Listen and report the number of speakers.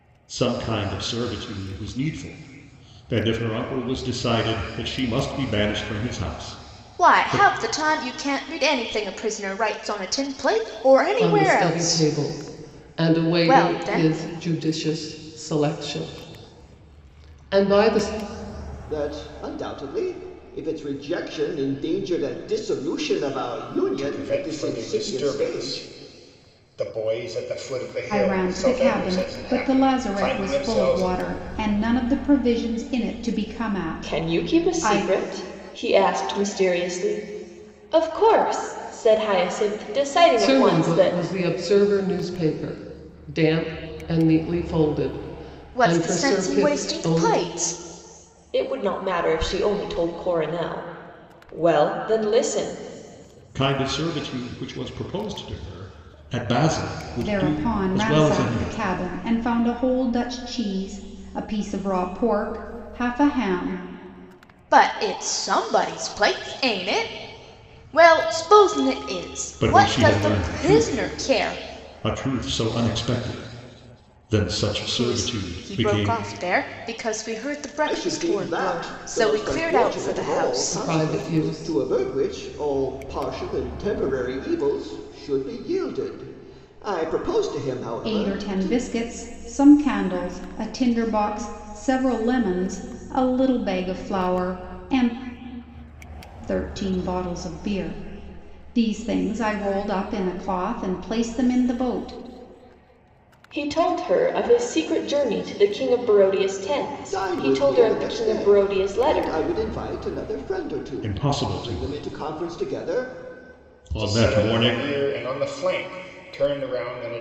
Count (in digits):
7